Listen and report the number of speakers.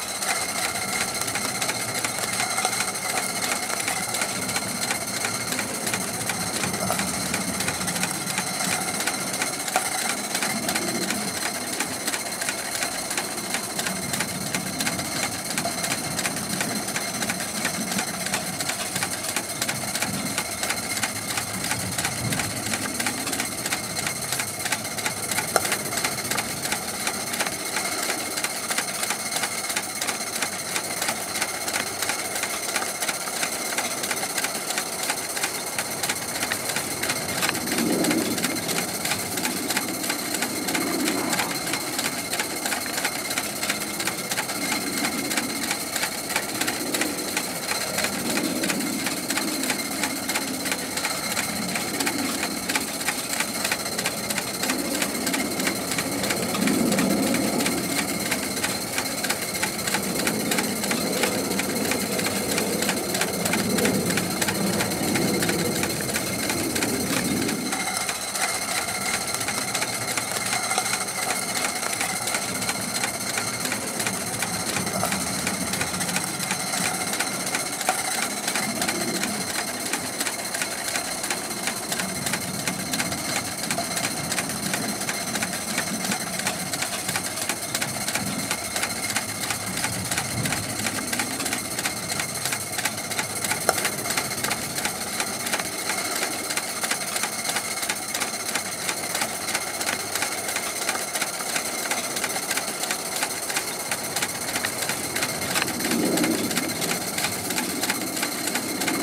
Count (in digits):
0